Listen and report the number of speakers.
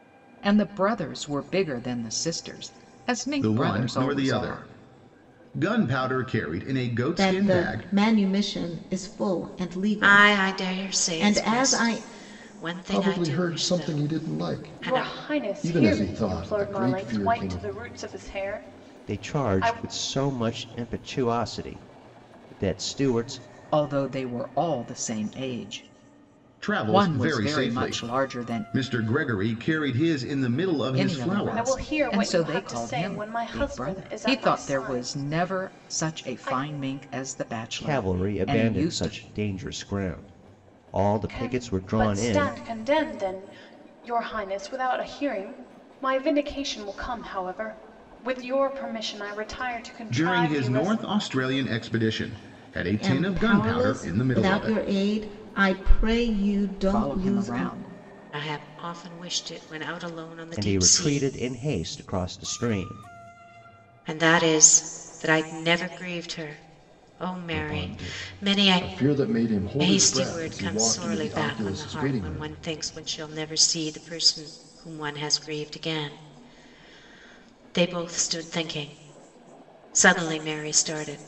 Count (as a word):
seven